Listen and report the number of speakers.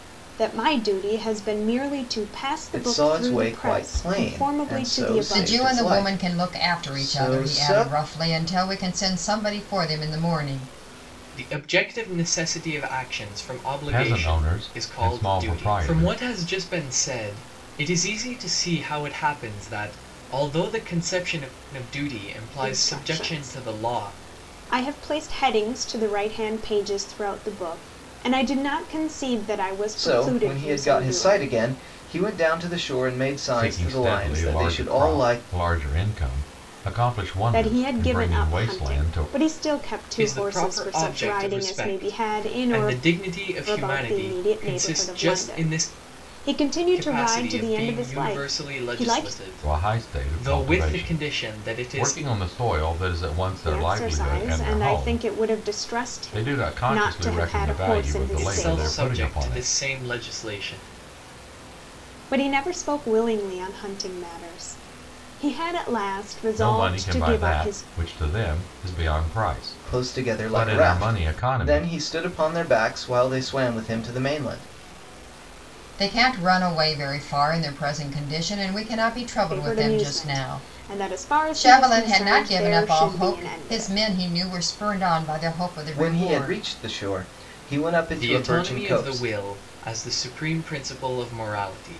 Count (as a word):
five